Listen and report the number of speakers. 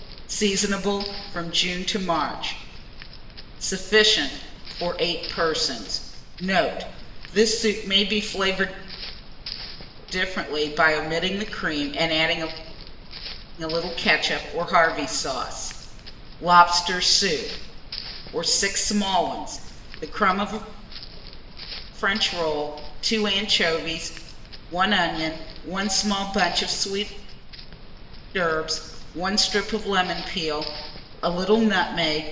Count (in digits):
1